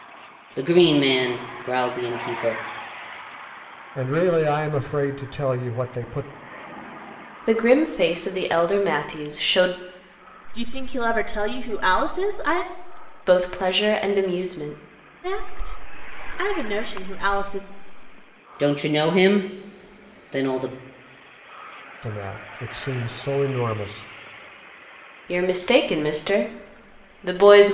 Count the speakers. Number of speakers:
4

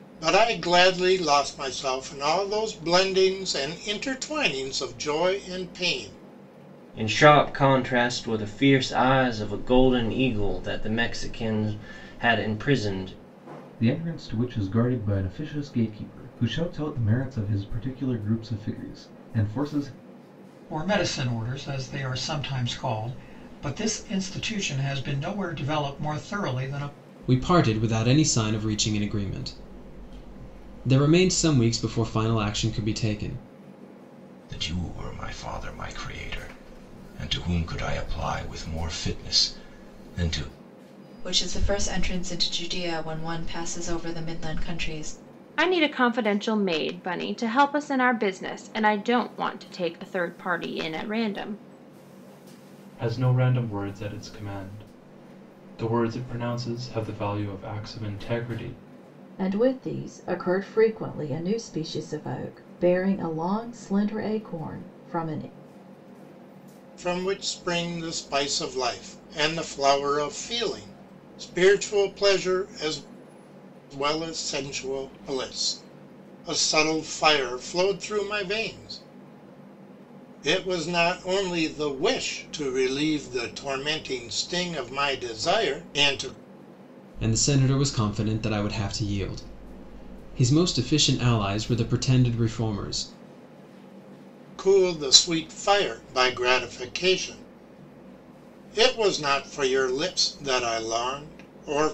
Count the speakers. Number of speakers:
10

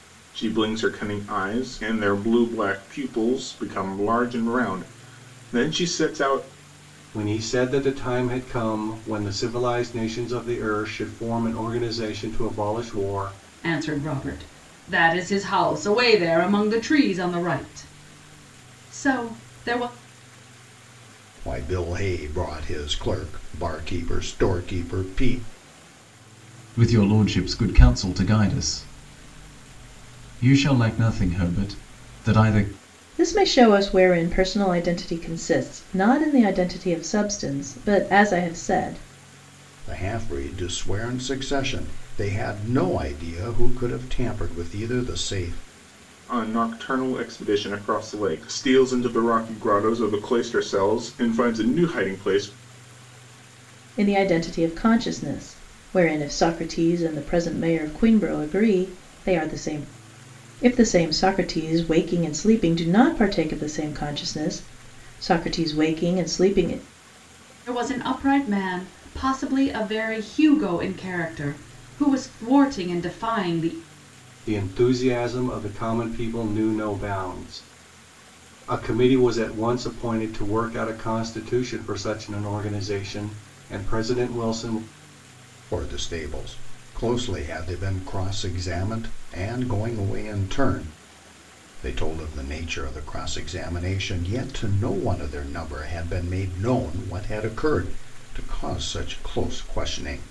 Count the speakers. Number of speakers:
6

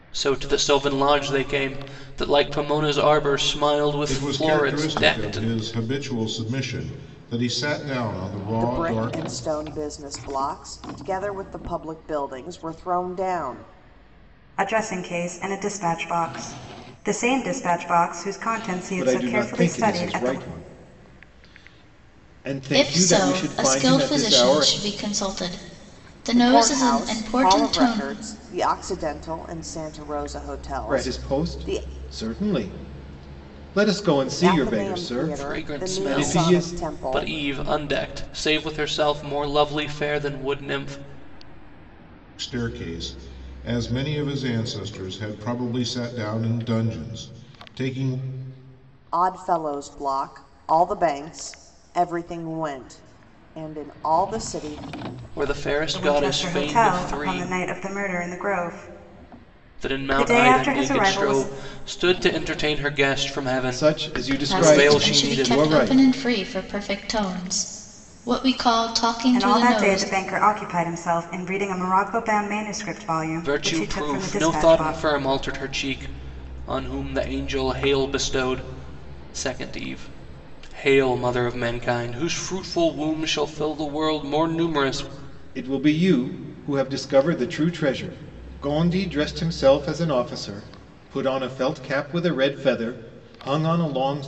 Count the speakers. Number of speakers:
6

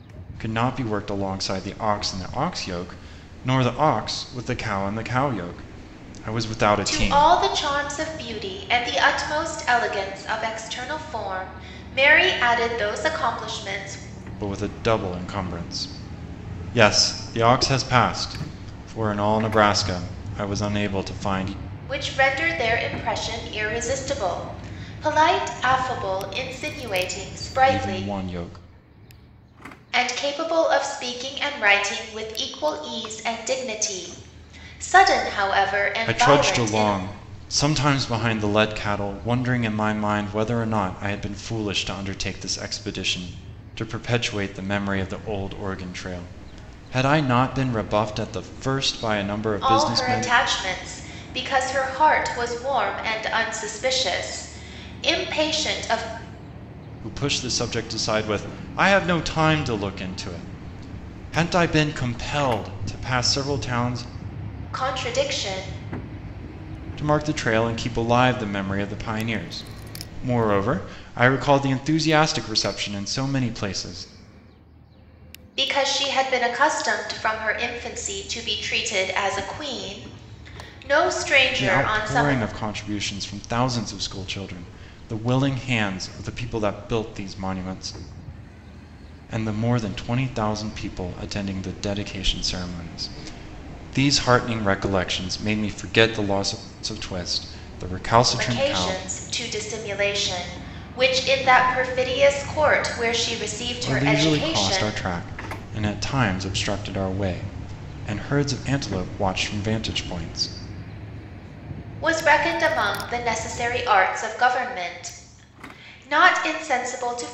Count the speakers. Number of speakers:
2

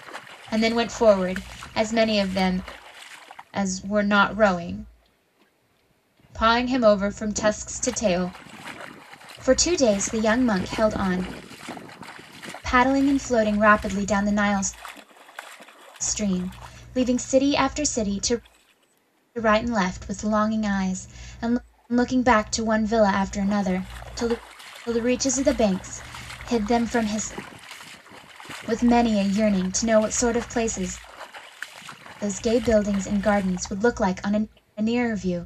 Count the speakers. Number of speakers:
1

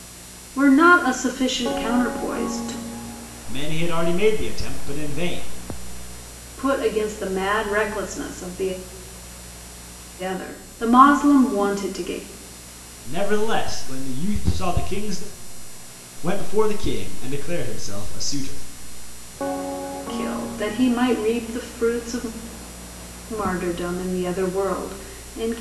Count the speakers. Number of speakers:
2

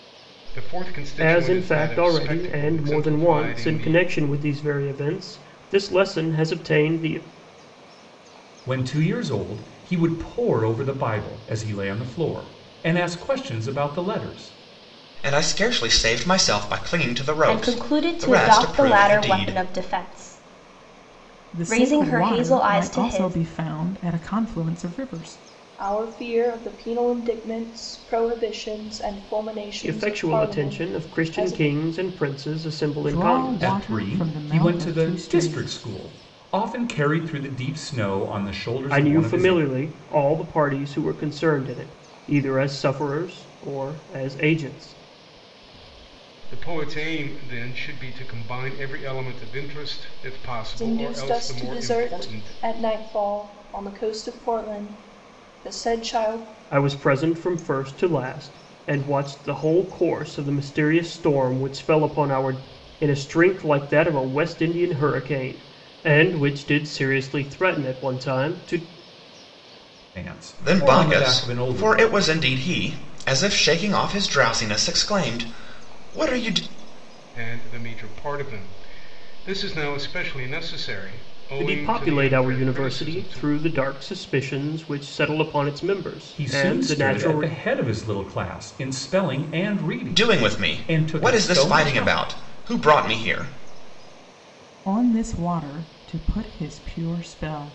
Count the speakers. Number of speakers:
7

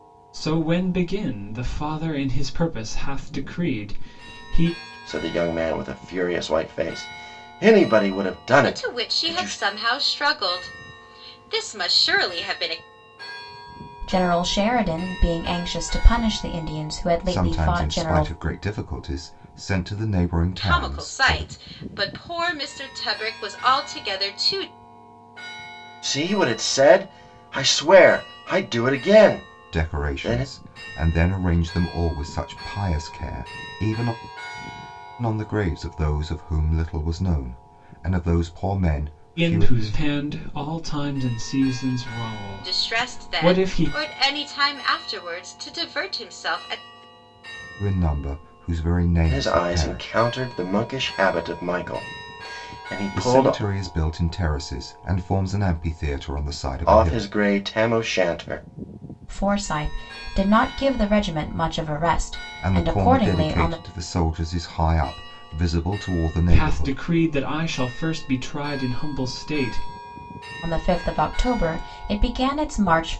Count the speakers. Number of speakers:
5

